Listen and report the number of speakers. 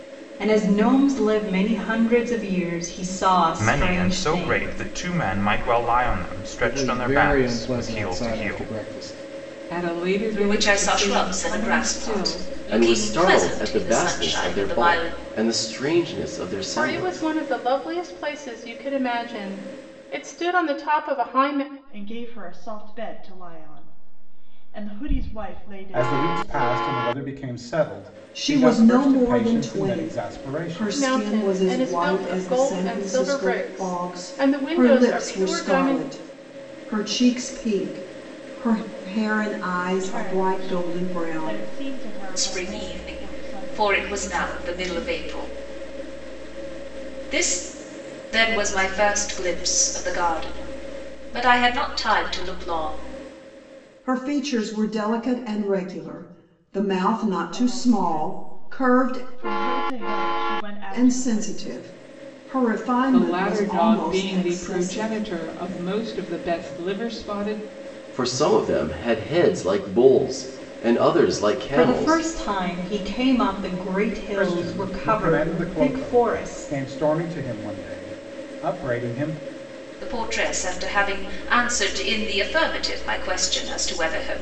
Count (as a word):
ten